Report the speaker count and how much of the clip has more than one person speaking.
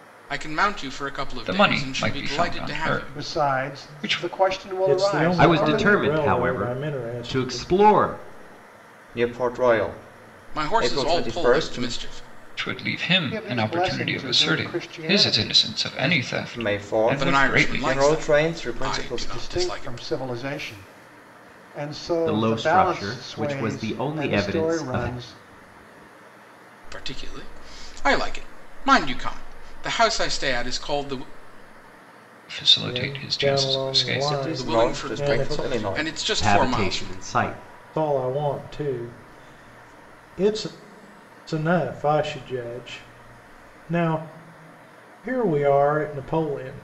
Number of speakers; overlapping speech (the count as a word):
six, about 43%